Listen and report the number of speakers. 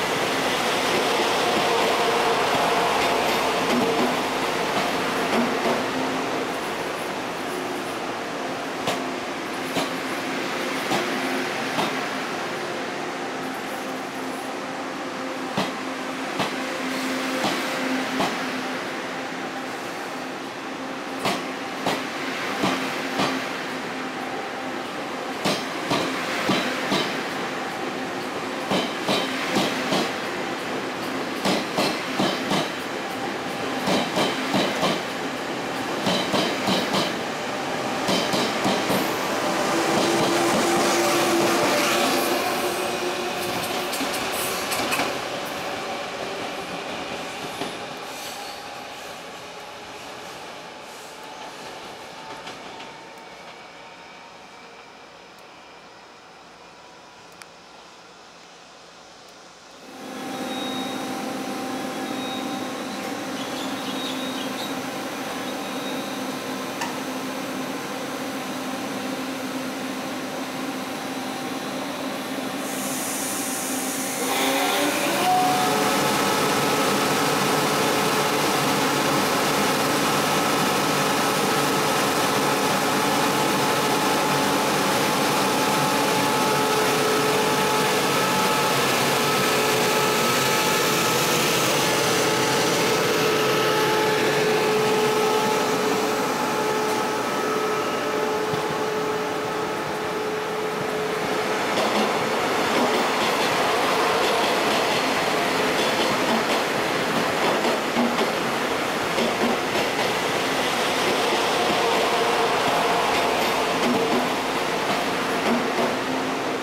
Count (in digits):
0